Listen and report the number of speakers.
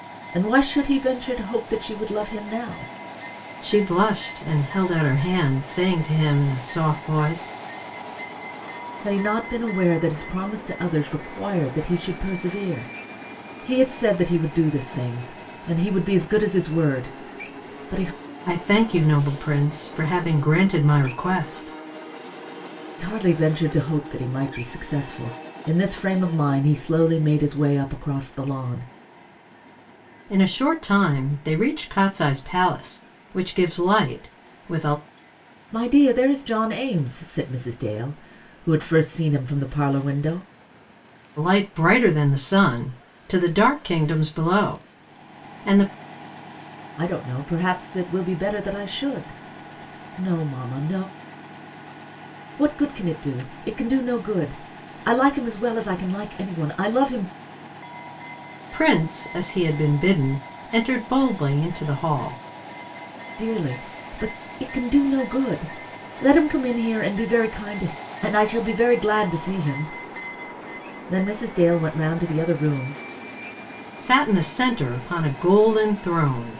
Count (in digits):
2